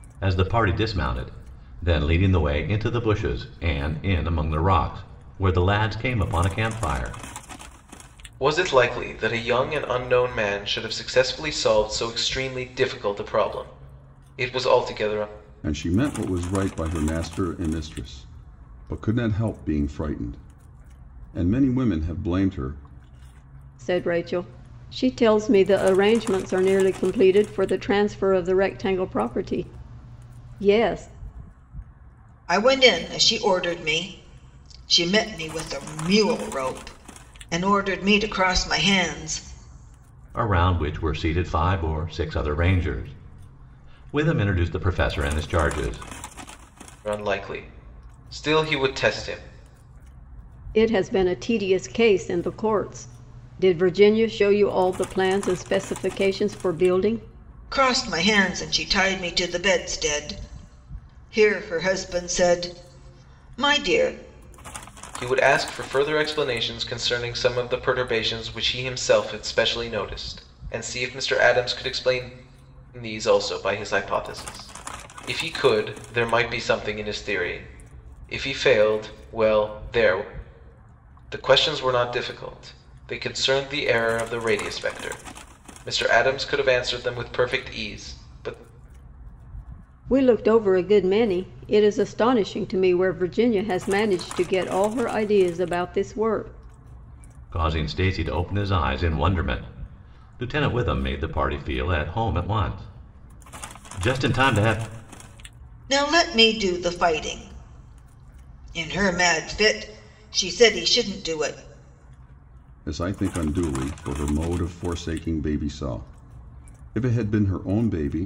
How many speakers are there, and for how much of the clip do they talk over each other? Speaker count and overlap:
5, no overlap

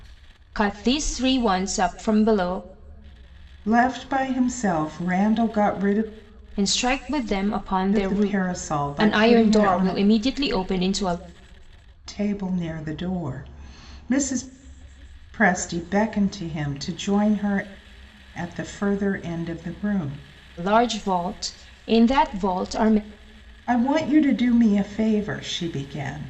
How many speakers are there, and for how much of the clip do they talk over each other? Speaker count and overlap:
2, about 6%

